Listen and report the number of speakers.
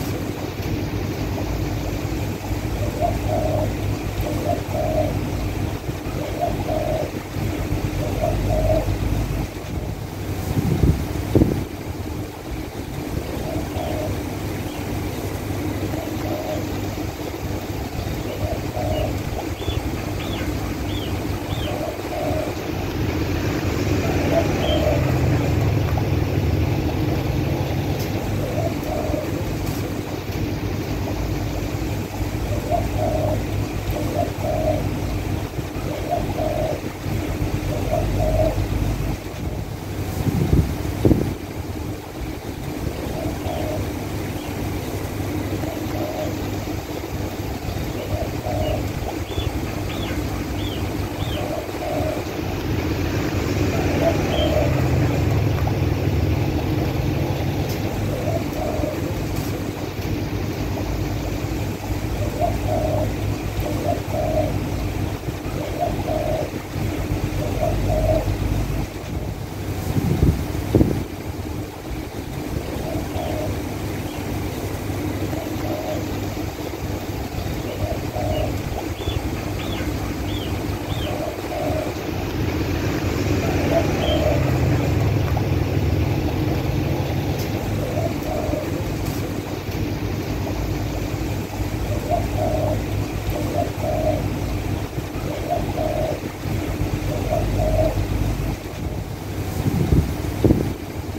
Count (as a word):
zero